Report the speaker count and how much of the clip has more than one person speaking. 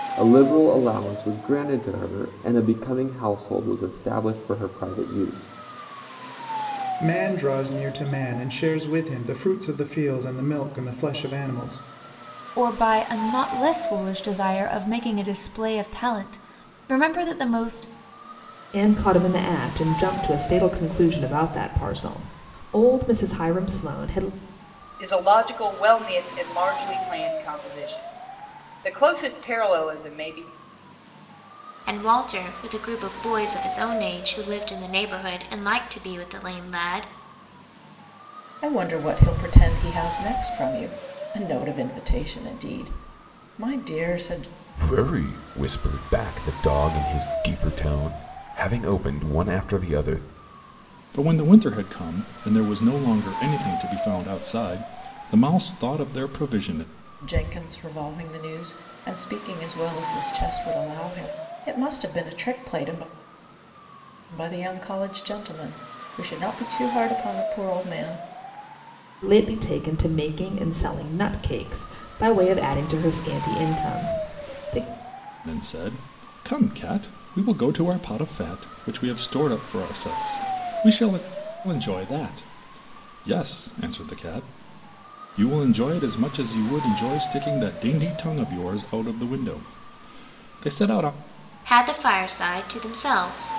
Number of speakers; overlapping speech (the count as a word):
nine, no overlap